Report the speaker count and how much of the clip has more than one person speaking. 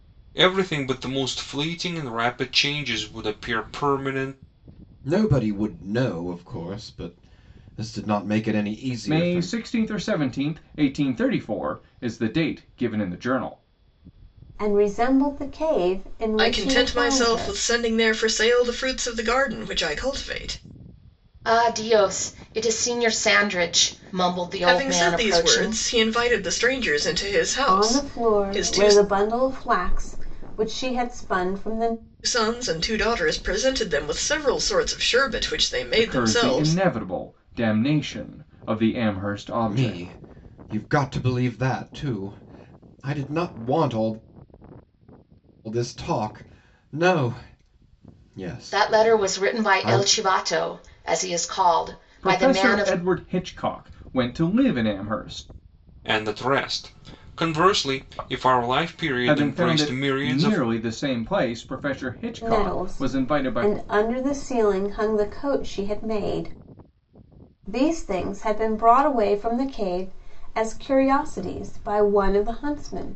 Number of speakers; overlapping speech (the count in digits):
6, about 14%